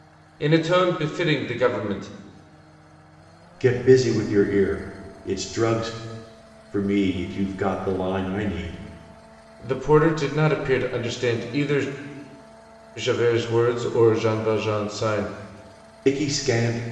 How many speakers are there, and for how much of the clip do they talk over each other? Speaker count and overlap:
2, no overlap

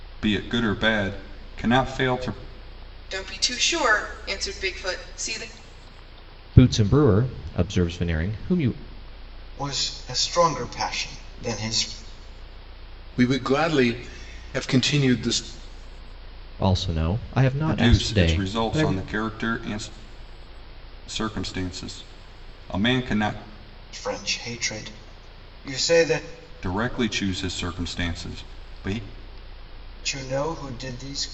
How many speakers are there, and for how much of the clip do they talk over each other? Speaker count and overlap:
5, about 4%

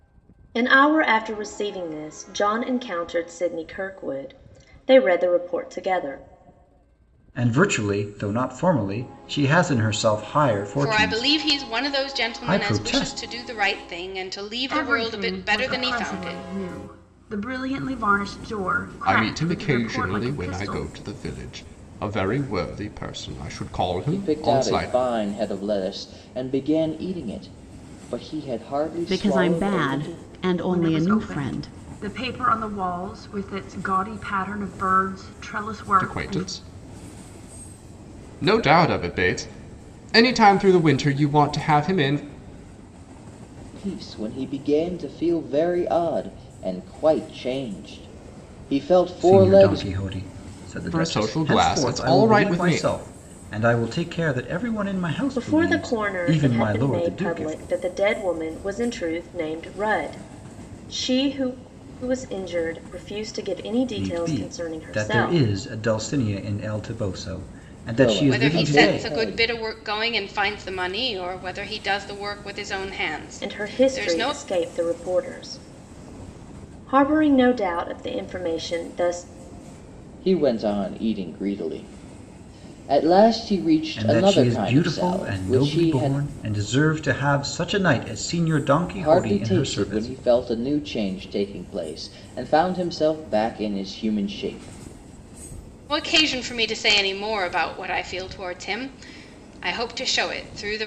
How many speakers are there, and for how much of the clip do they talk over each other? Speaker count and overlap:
7, about 23%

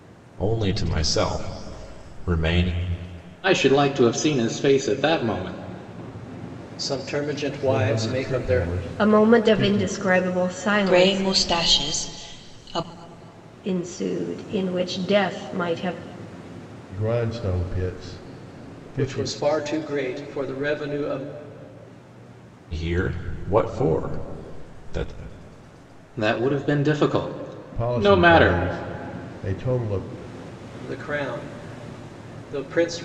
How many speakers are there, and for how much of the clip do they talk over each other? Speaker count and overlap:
6, about 12%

